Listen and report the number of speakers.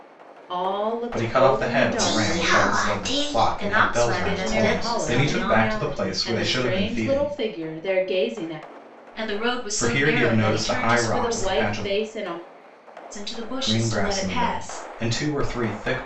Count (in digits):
3